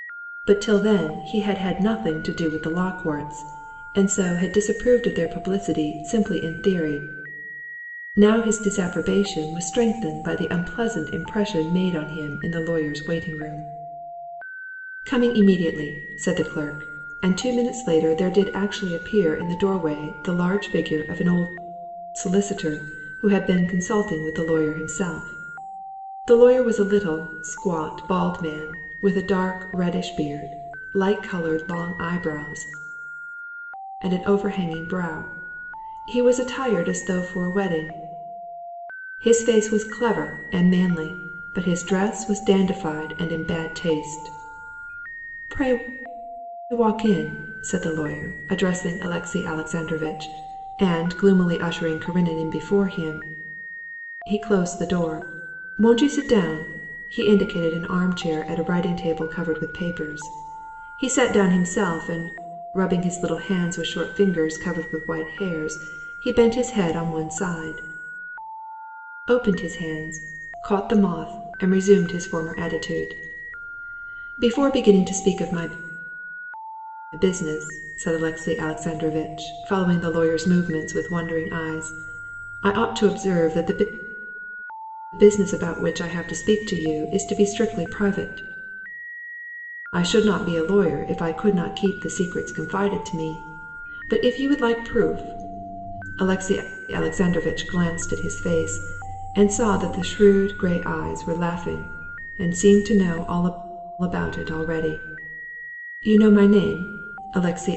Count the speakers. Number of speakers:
1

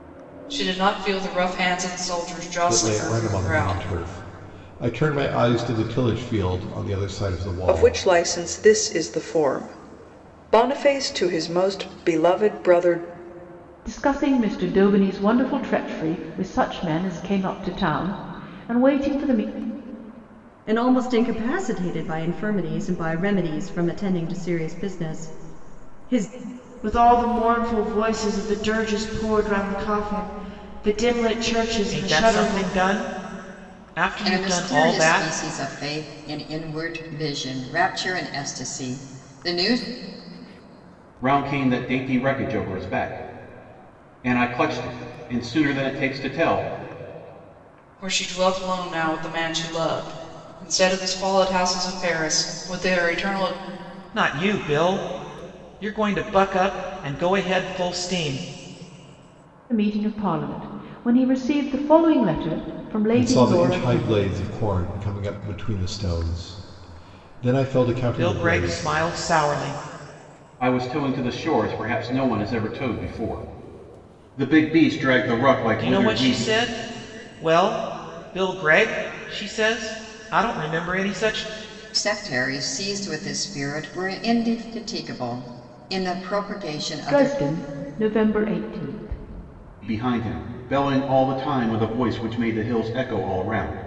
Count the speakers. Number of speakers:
9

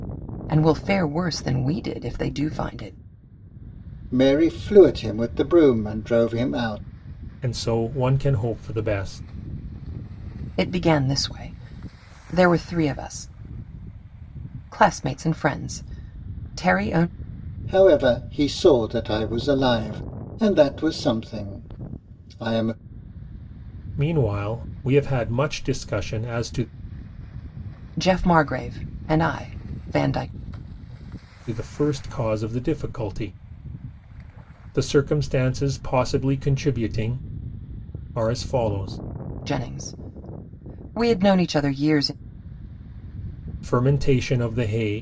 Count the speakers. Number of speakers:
3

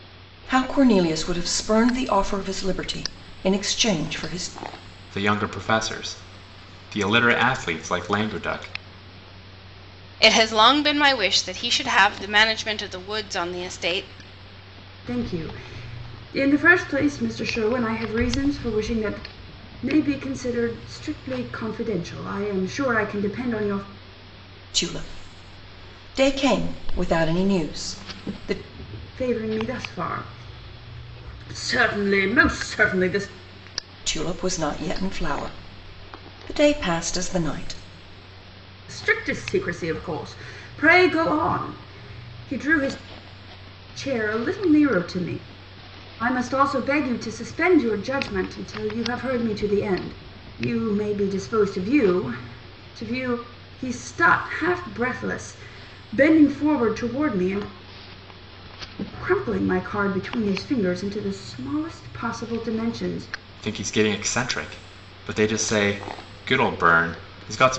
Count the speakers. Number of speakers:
4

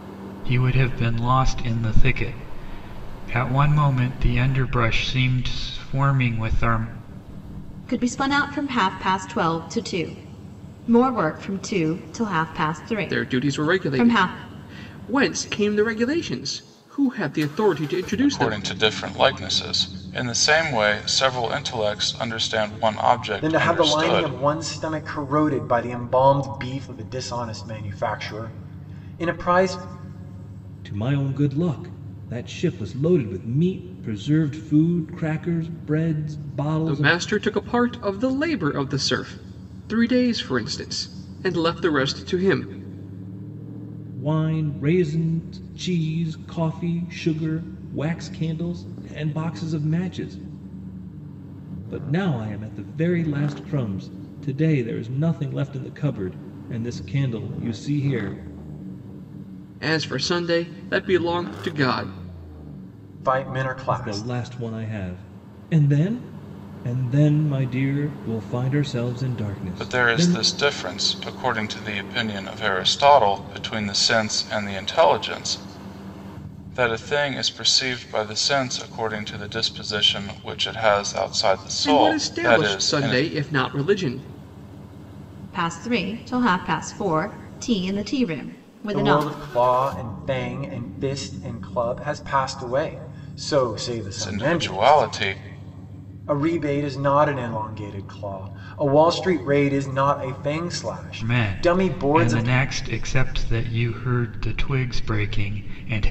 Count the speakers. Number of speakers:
6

